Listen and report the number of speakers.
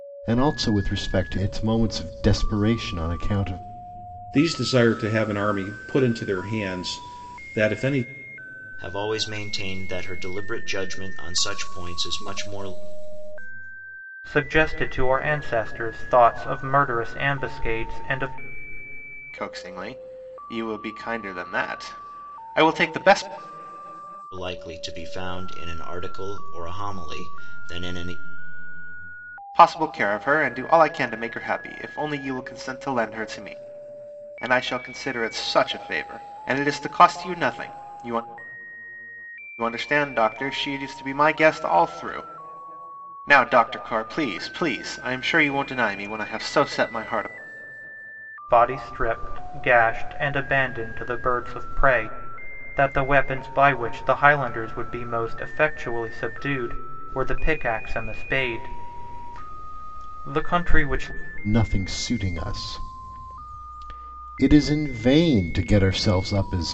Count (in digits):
5